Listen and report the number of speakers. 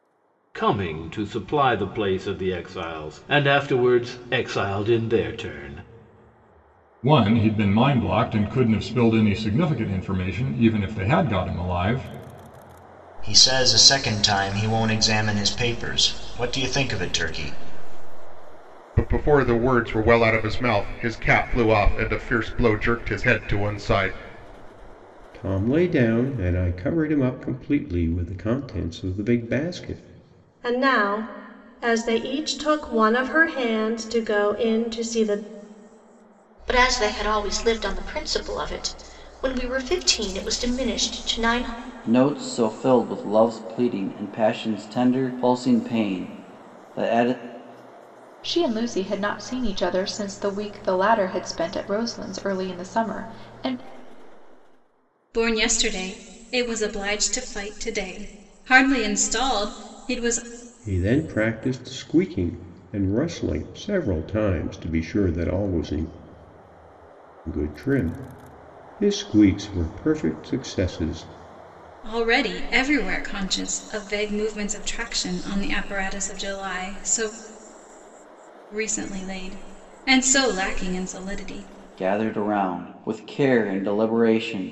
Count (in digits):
10